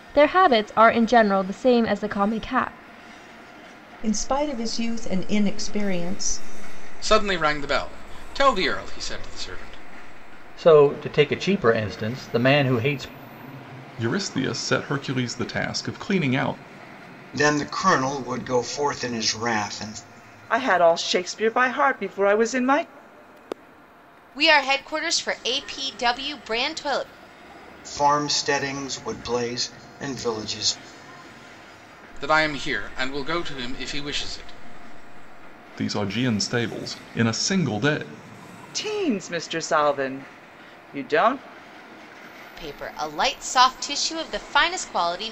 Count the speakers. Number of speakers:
eight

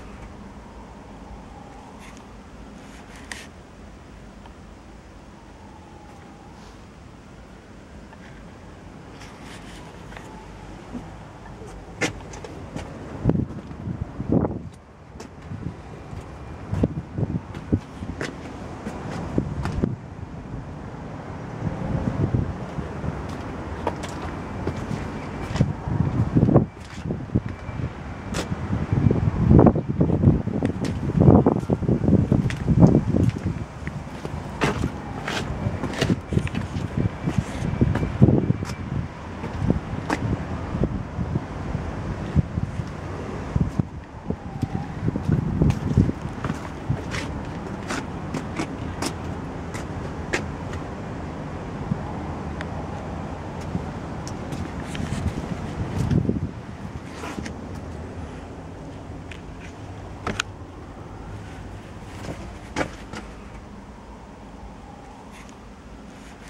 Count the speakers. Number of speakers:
zero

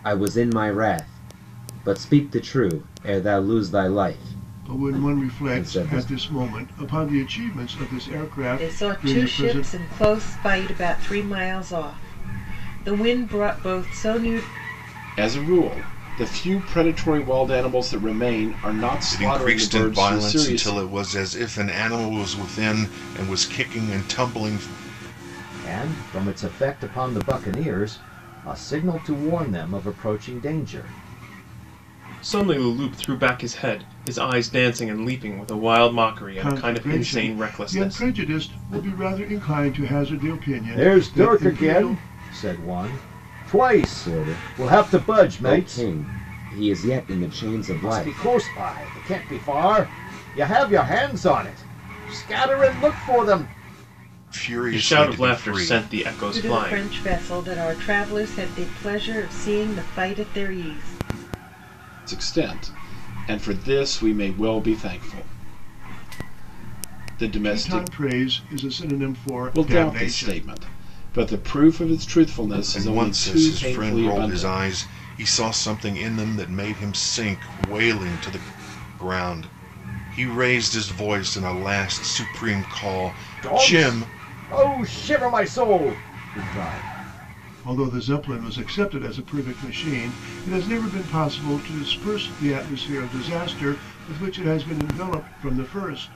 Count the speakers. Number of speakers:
seven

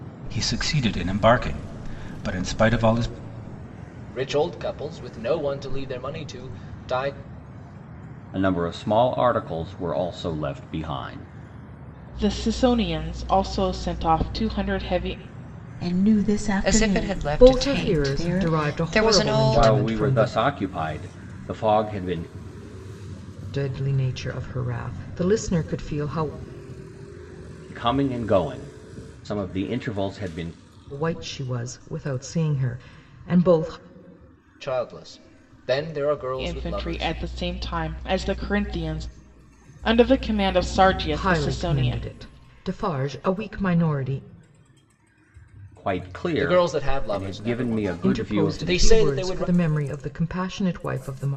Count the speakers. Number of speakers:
seven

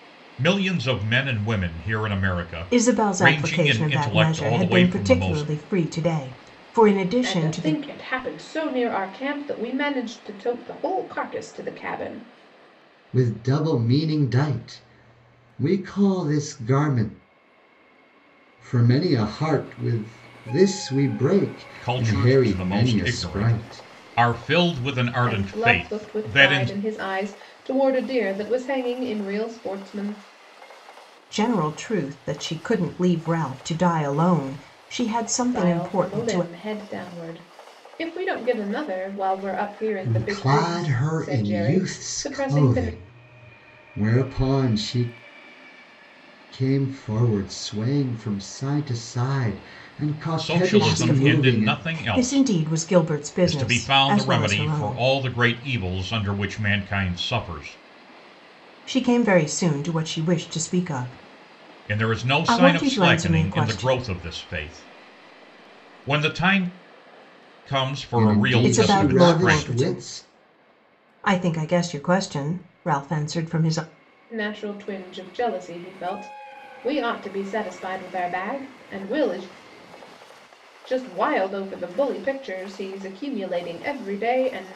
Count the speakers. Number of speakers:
four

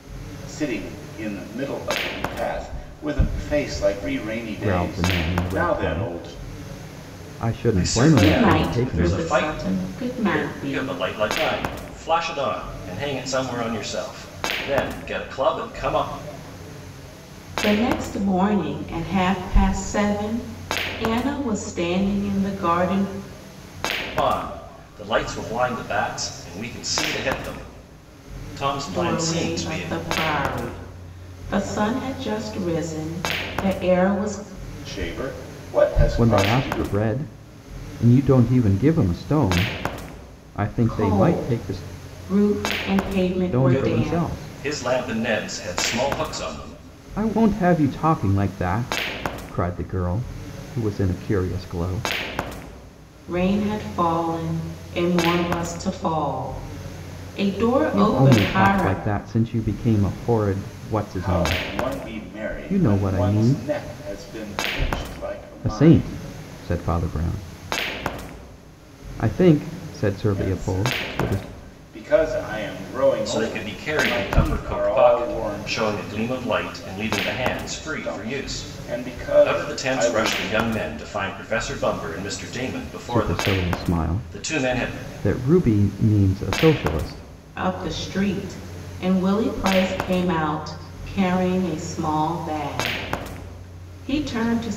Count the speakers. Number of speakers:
four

